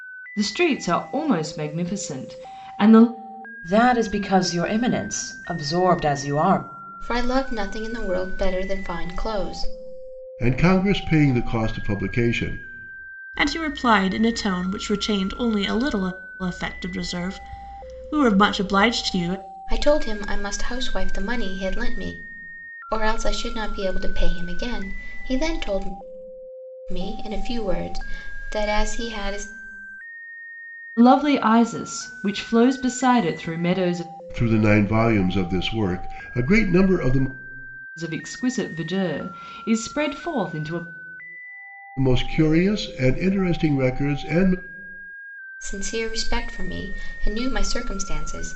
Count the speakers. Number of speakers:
five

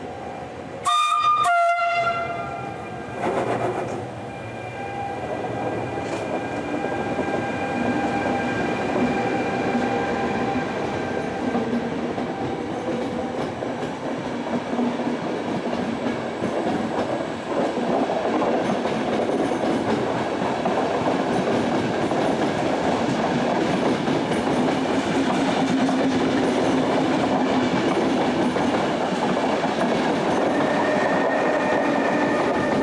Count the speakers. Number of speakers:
zero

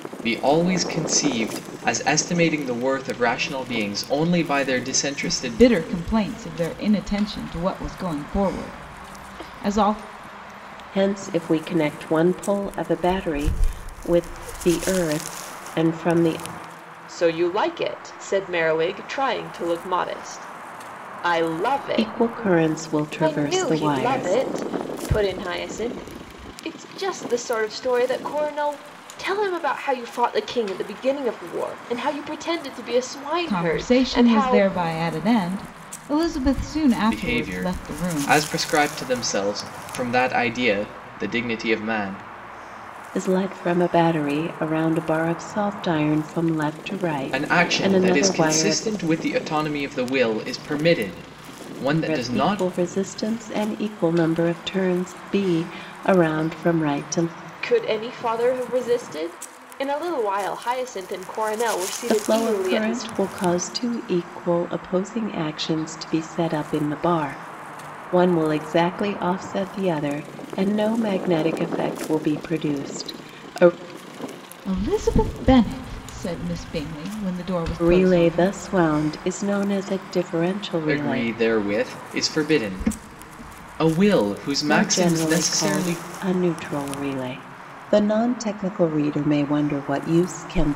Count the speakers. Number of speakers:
four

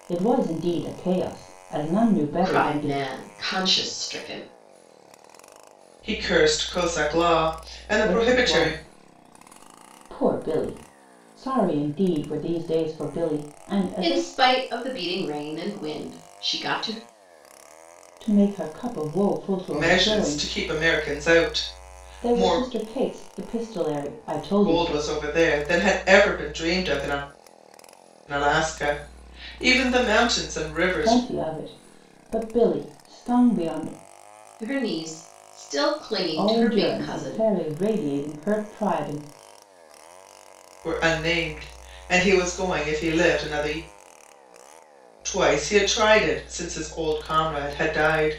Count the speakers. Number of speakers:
three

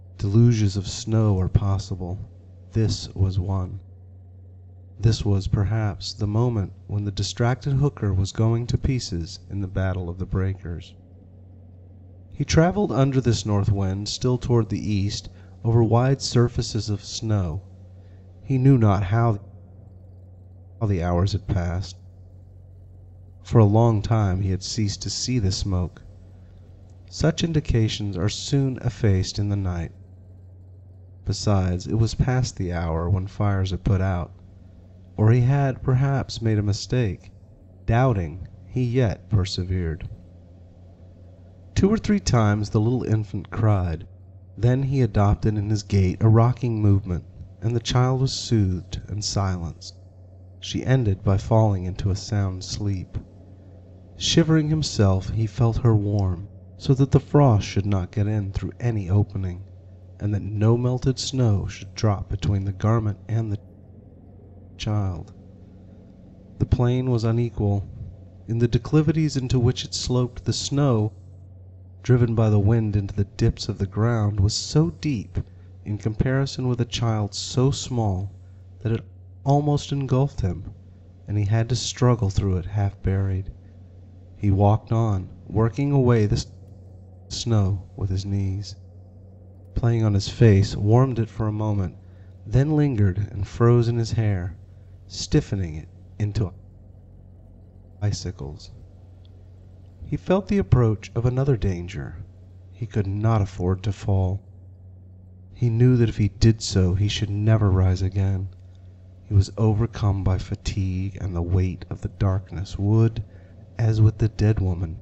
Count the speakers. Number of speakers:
one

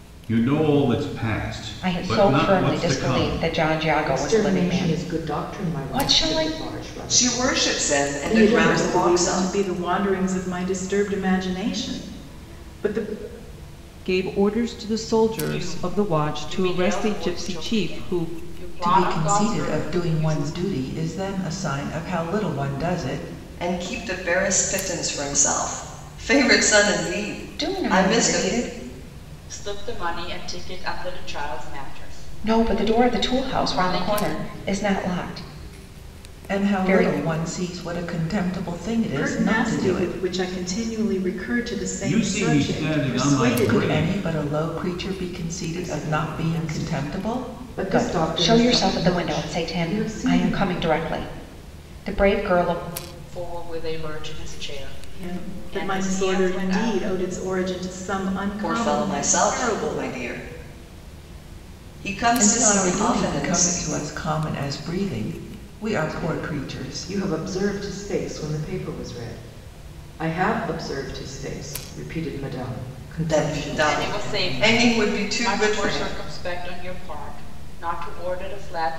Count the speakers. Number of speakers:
eight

